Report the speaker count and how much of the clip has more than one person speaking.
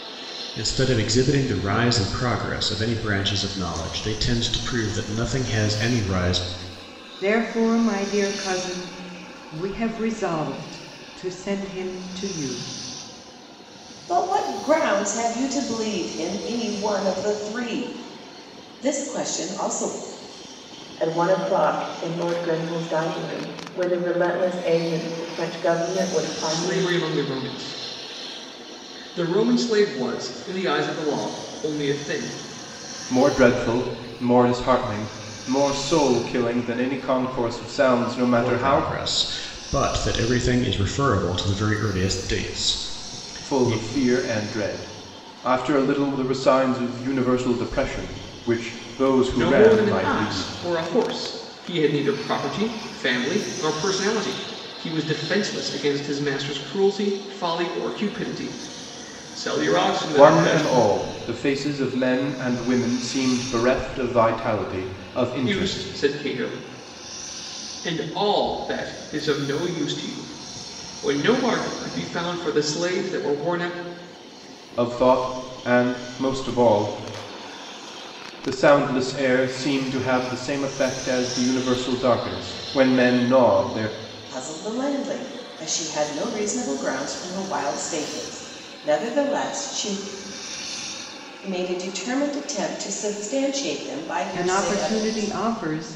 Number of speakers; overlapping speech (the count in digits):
6, about 5%